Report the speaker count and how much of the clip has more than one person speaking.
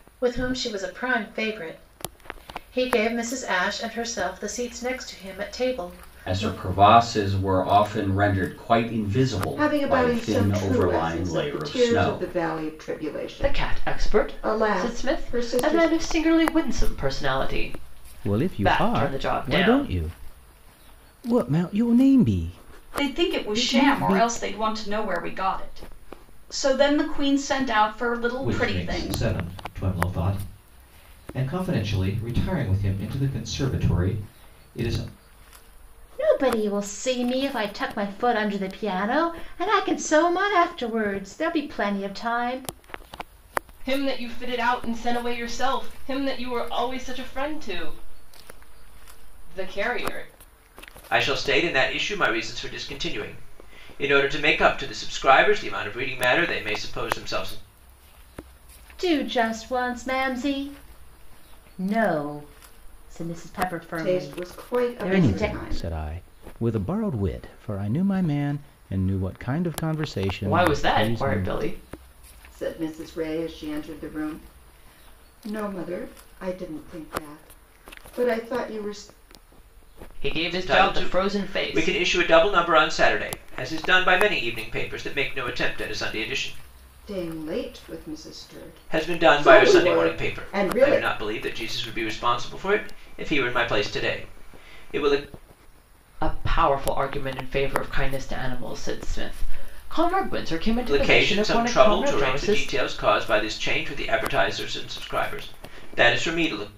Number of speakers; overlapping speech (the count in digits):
10, about 17%